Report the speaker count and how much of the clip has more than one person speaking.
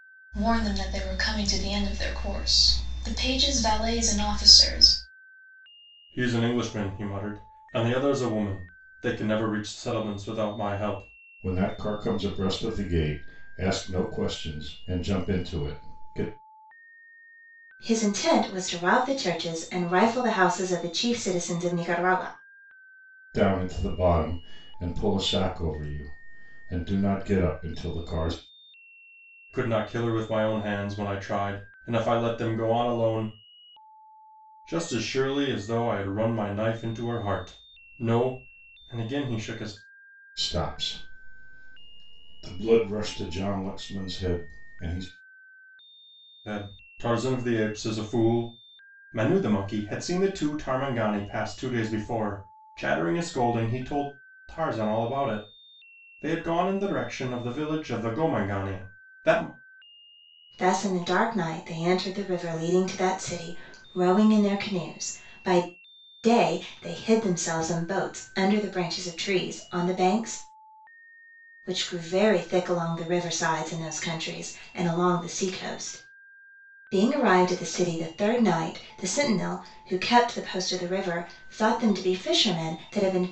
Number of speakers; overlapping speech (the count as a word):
four, no overlap